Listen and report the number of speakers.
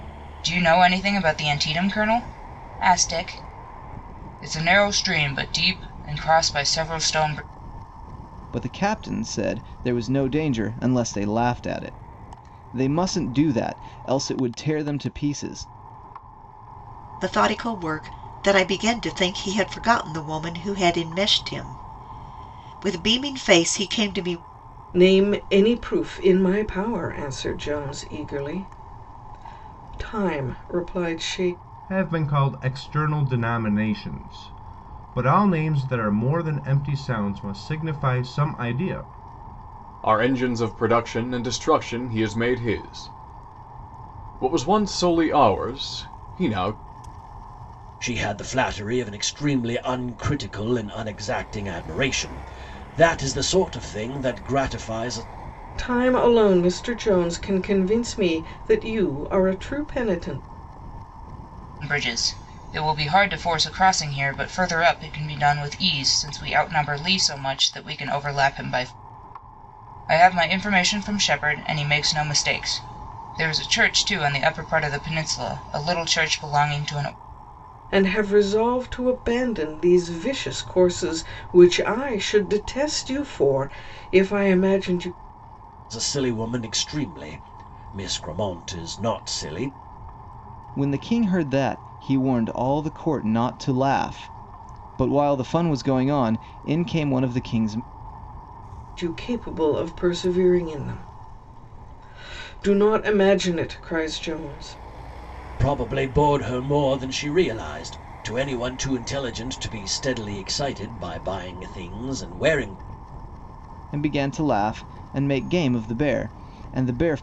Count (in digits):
7